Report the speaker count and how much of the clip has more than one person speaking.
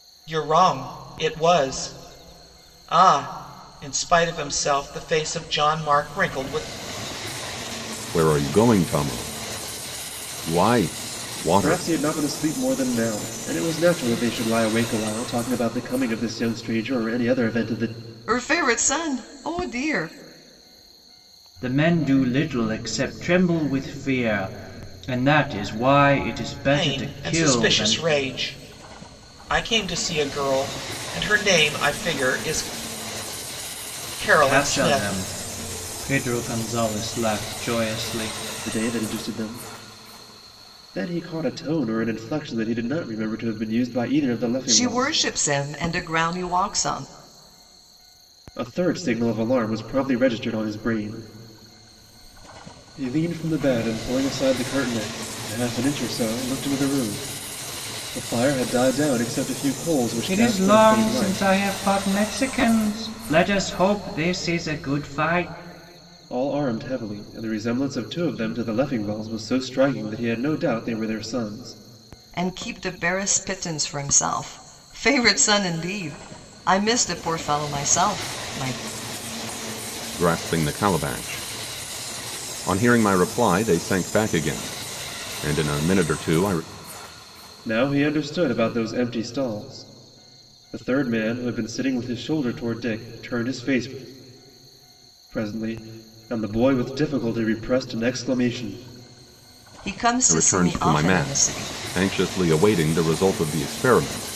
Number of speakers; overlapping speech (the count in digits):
5, about 6%